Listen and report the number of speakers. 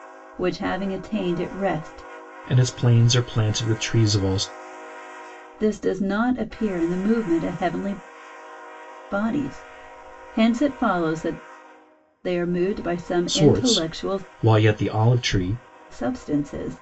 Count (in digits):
2